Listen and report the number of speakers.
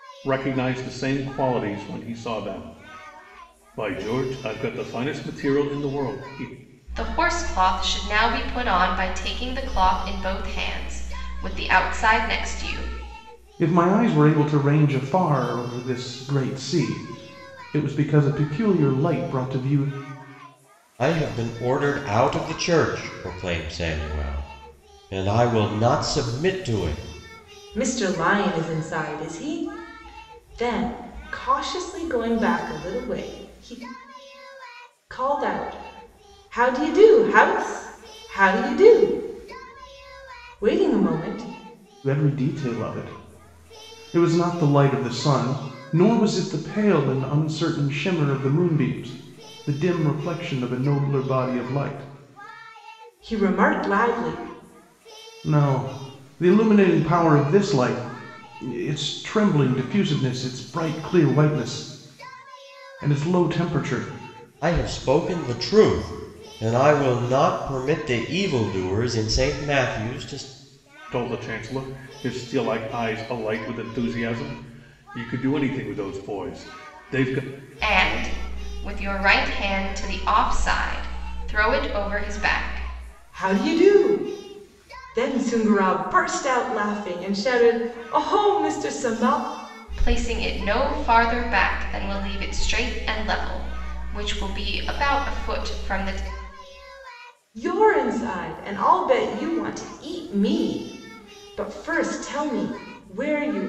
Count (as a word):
five